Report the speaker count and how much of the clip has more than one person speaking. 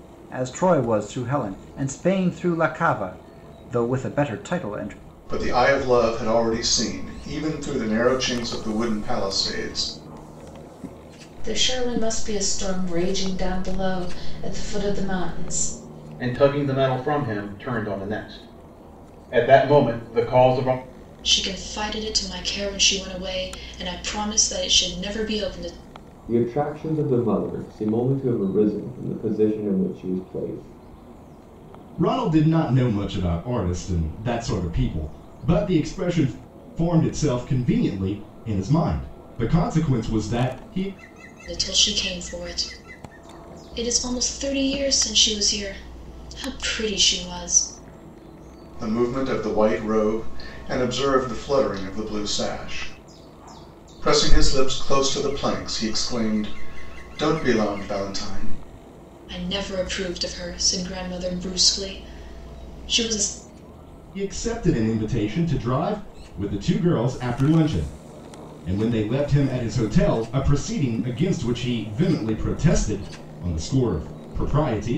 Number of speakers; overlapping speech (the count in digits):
7, no overlap